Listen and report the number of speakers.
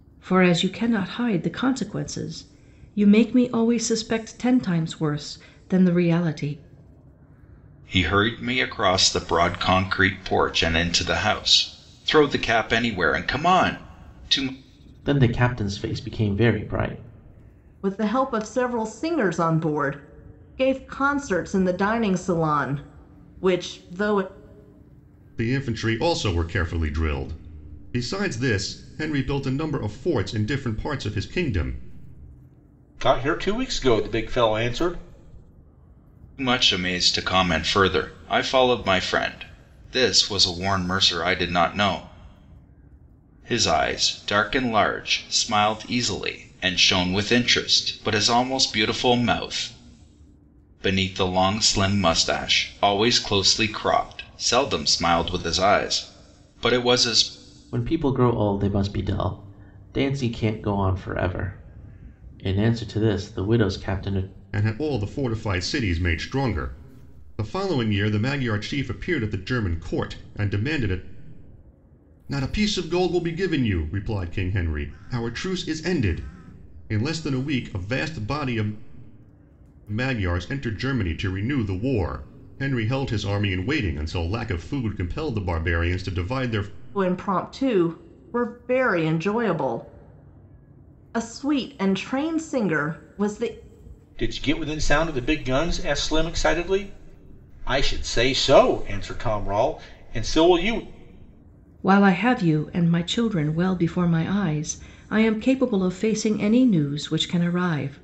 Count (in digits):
6